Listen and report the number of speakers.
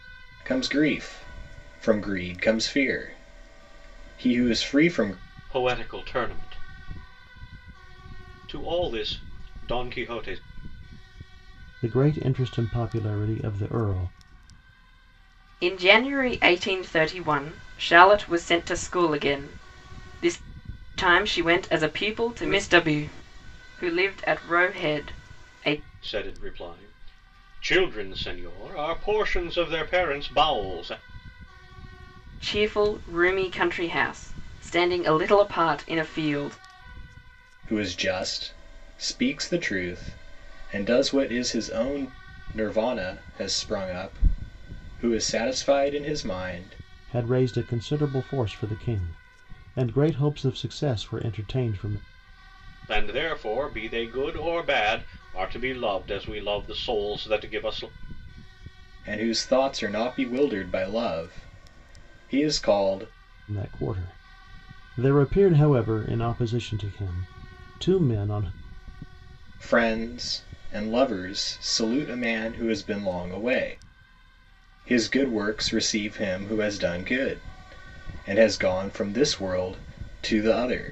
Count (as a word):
four